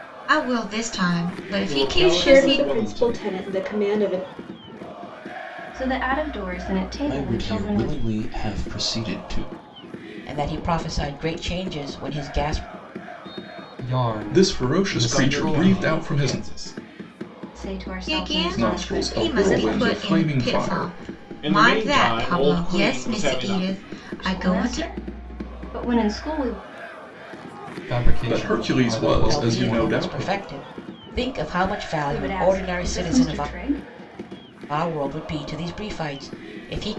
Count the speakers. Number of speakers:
8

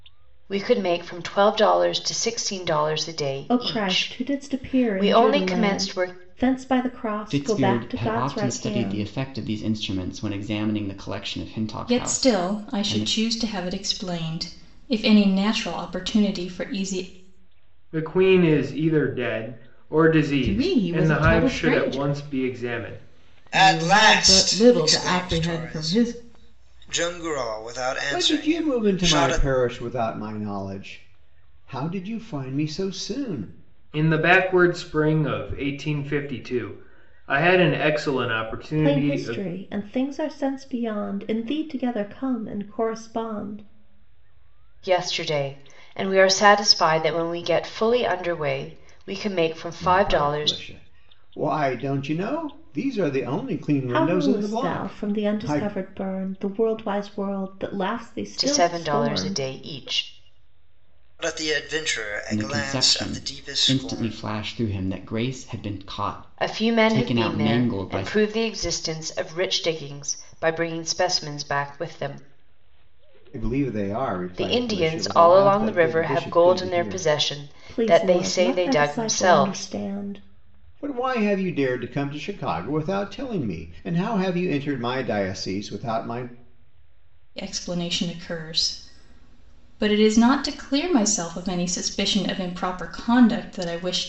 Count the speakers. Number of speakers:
8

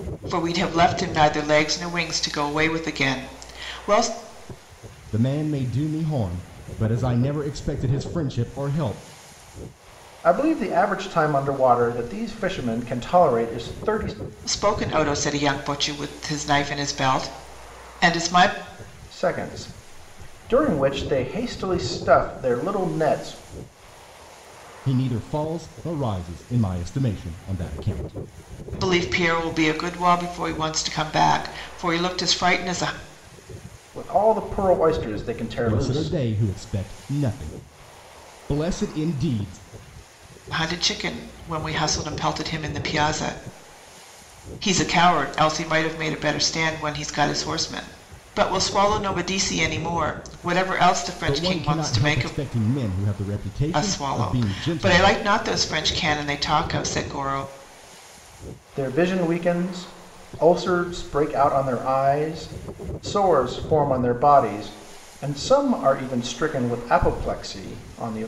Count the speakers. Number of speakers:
3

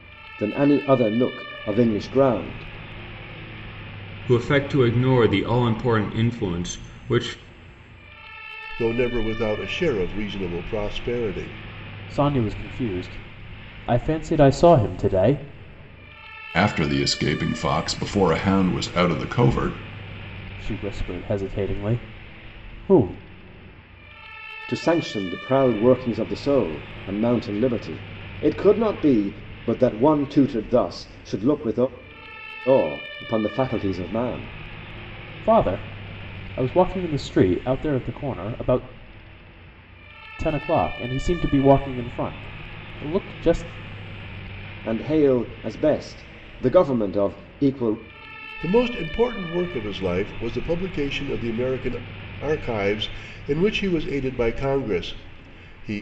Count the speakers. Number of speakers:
5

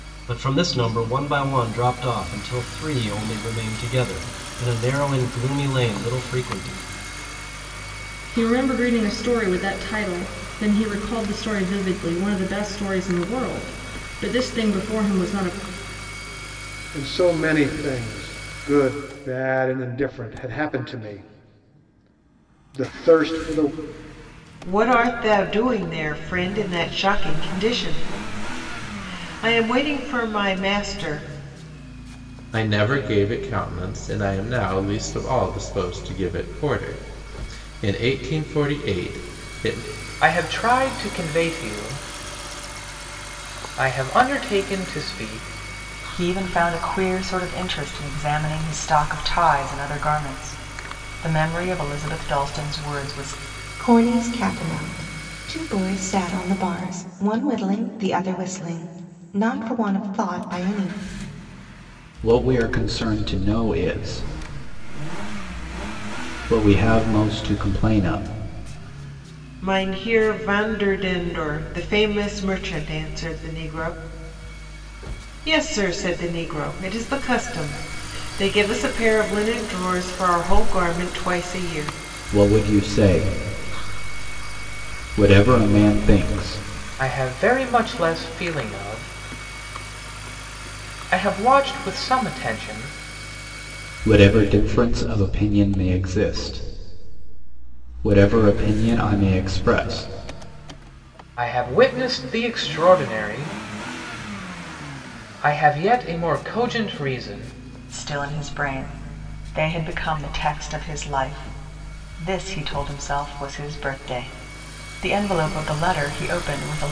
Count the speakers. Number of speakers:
9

